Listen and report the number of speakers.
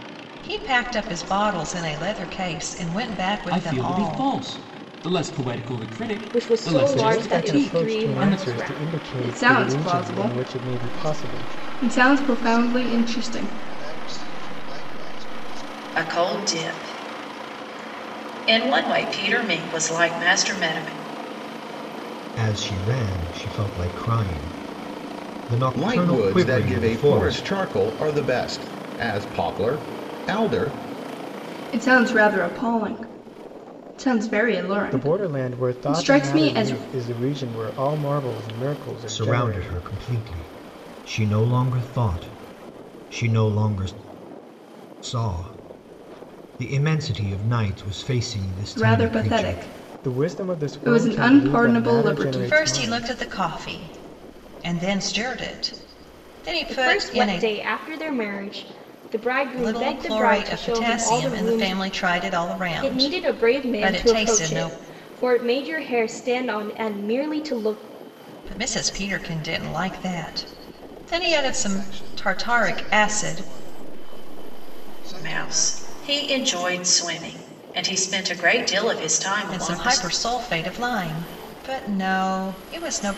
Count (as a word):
nine